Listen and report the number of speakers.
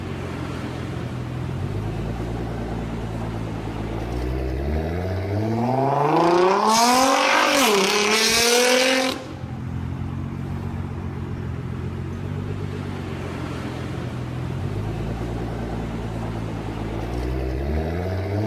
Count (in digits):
0